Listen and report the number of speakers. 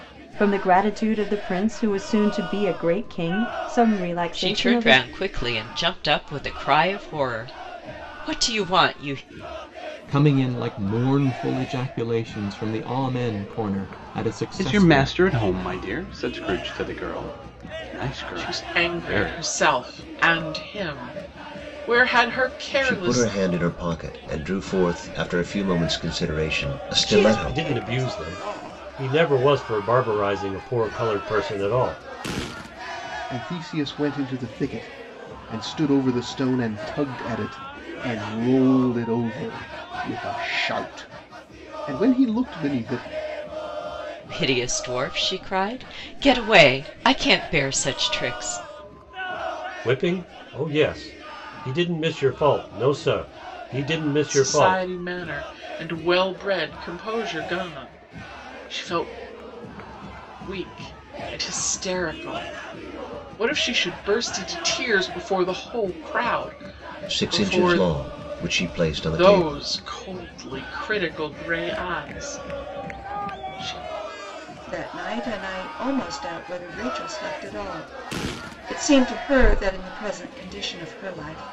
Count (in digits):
9